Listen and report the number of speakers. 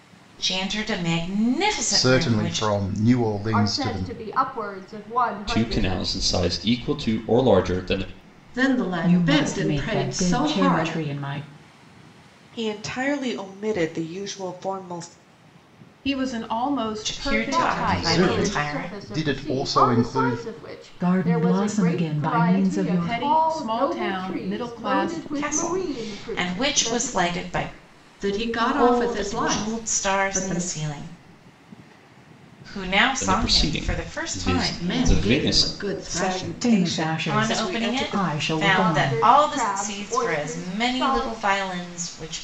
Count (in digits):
8